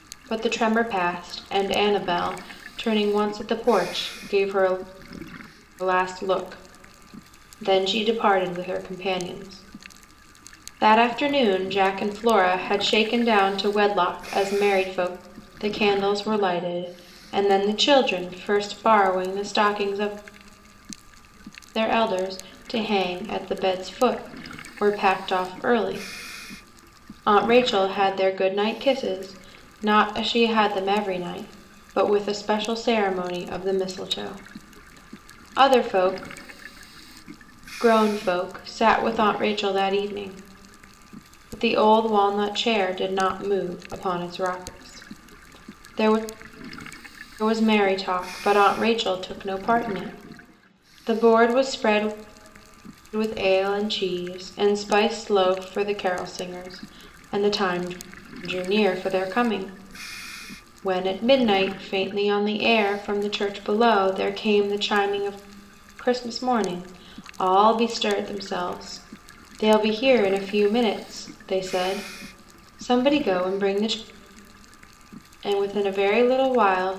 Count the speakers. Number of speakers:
one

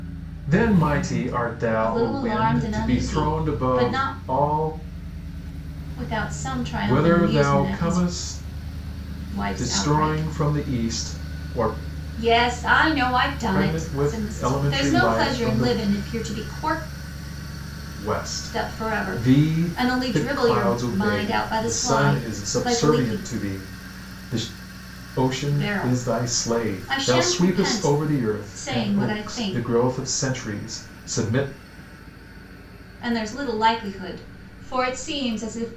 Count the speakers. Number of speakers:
two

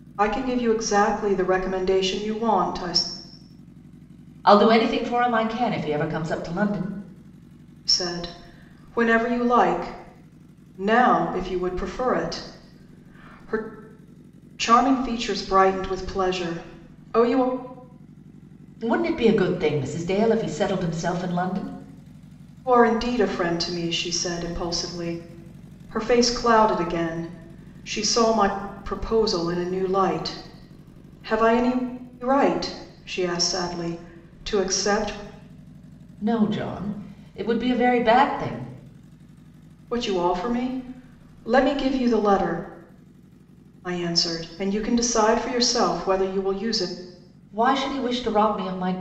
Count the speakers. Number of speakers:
two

